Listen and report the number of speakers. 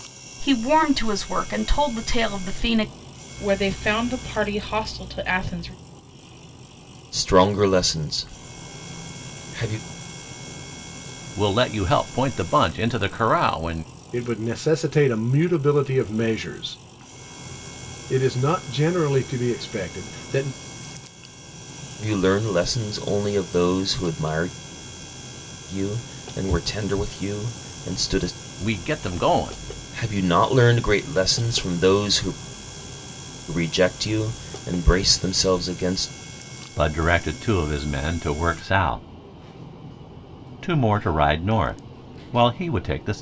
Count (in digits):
5